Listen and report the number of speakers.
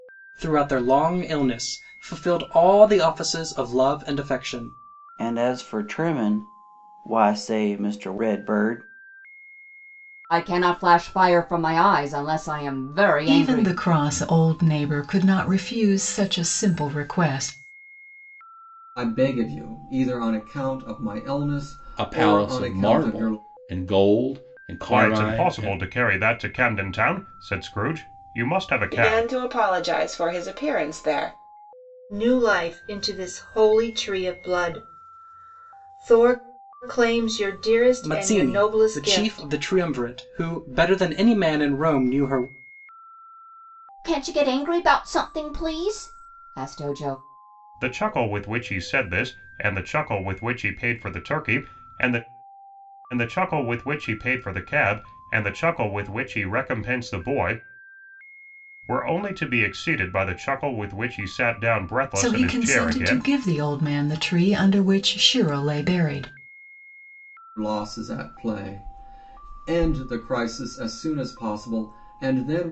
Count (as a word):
nine